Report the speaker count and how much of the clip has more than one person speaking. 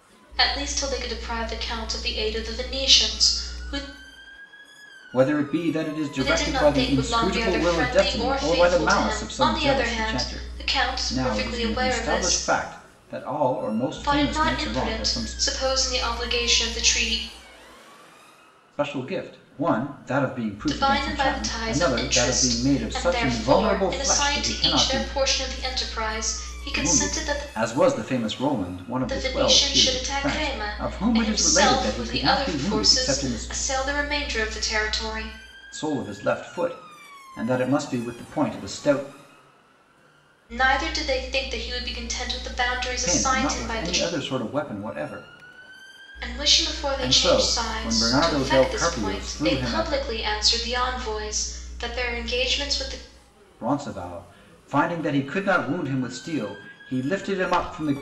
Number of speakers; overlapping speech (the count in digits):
2, about 37%